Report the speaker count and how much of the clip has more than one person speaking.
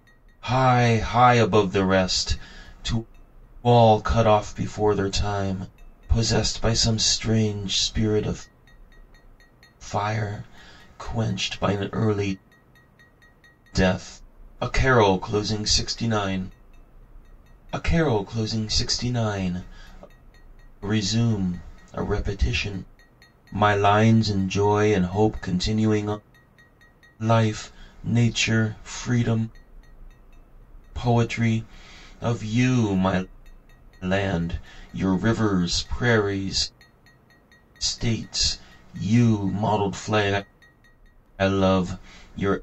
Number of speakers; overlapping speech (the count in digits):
1, no overlap